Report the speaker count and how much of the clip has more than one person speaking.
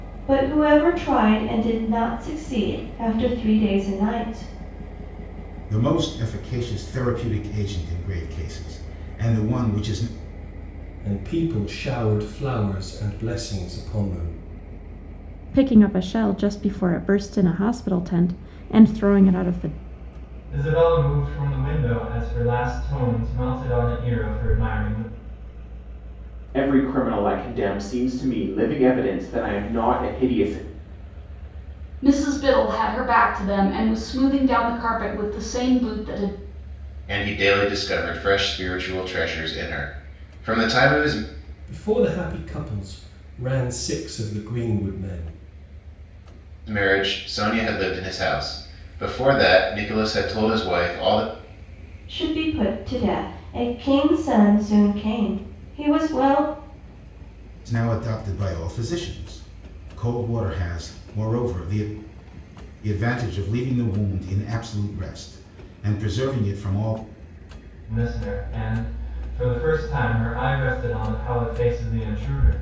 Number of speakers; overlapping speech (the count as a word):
eight, no overlap